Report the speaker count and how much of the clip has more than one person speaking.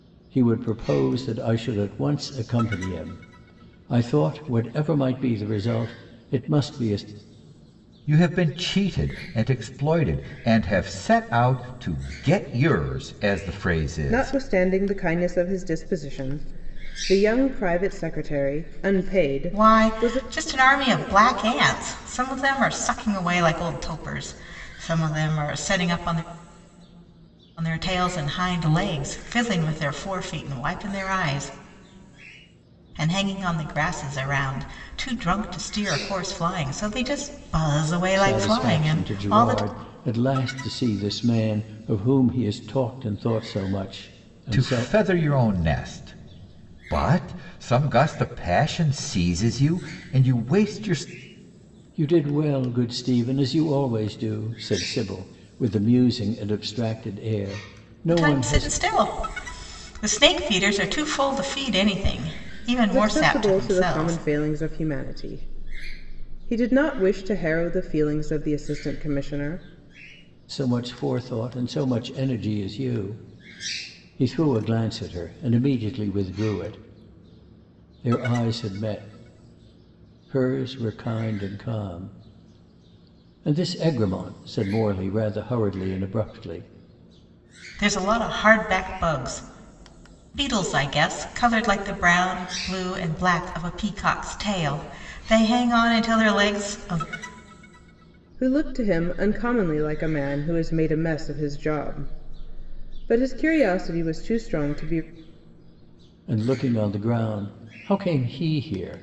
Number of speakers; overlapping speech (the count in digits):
4, about 4%